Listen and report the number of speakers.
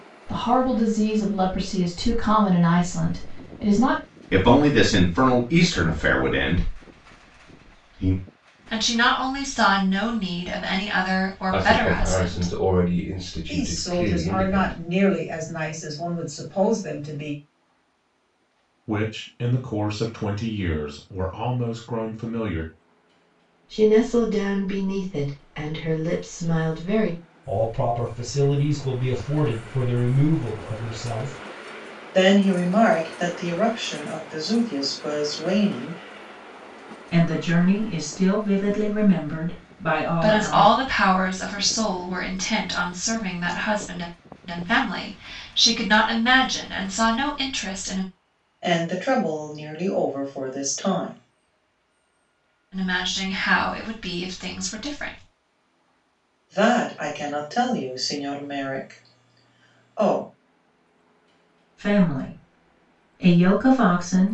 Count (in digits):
10